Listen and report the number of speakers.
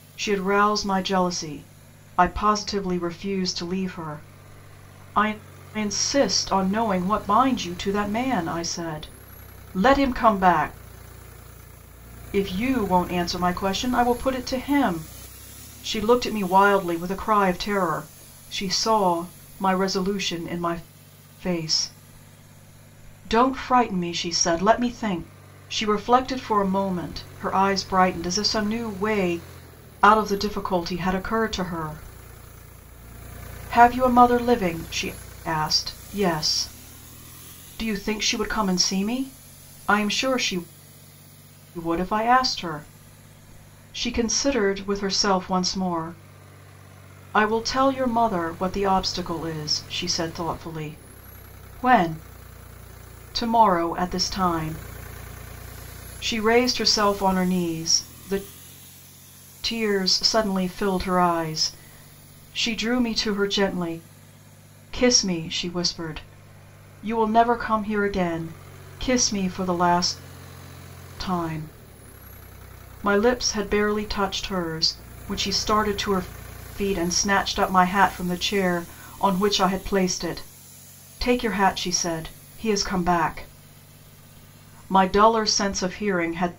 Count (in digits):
1